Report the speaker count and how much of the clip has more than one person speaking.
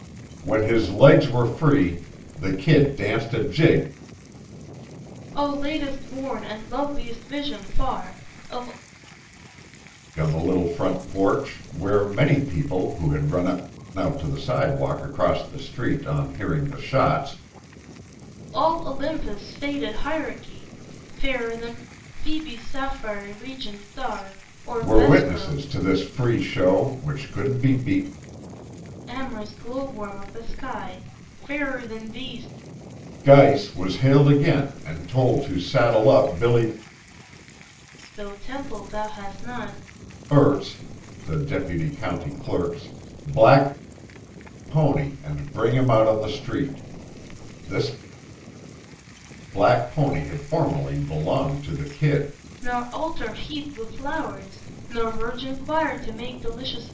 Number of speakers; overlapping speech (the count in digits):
2, about 1%